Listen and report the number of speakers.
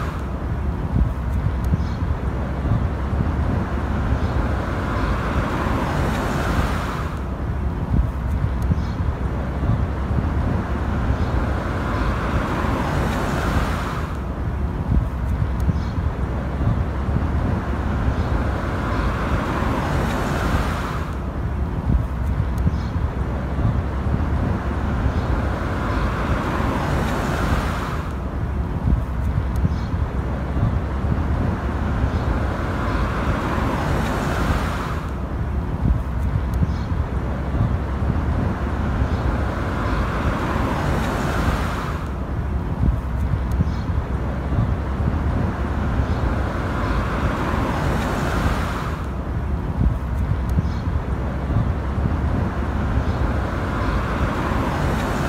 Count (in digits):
0